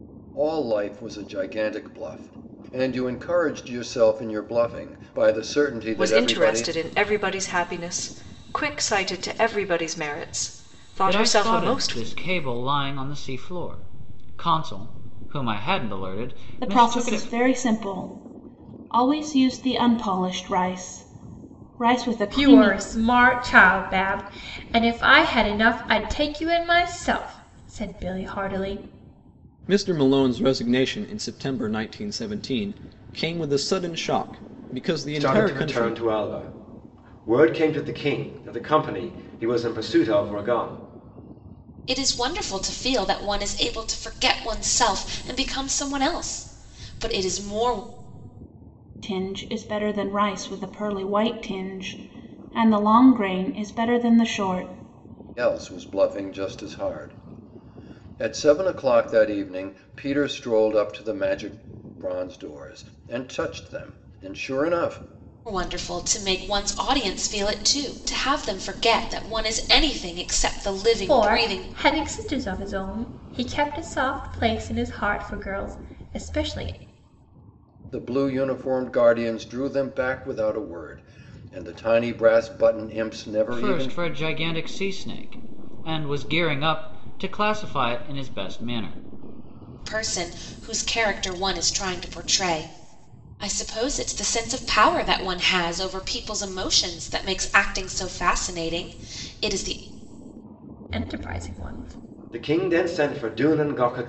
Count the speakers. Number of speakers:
8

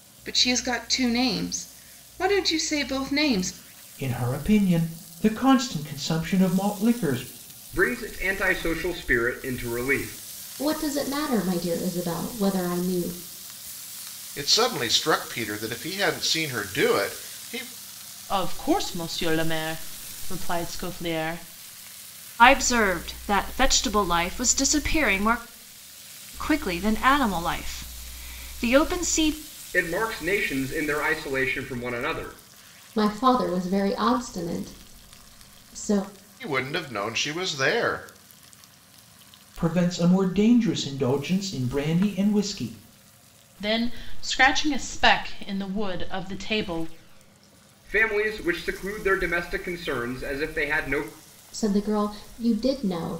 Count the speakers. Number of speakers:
7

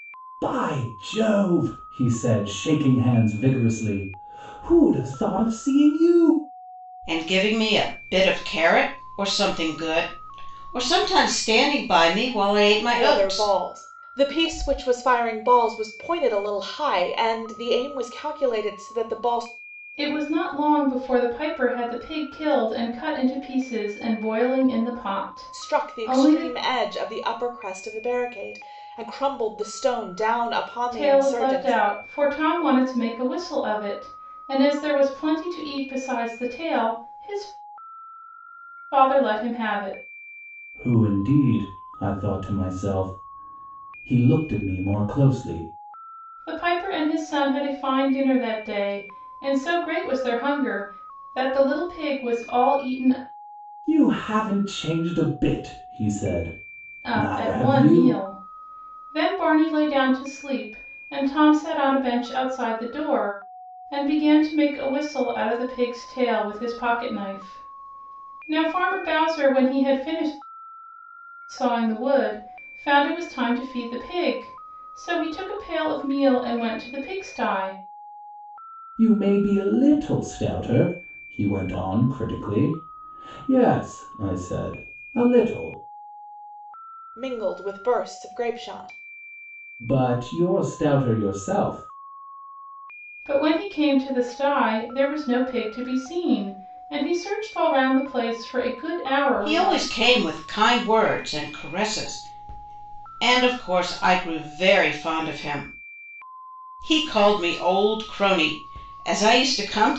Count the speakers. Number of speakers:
4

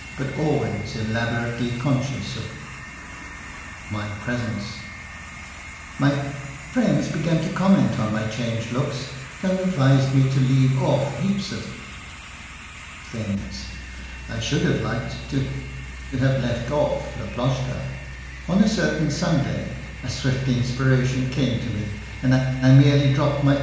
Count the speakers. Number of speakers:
1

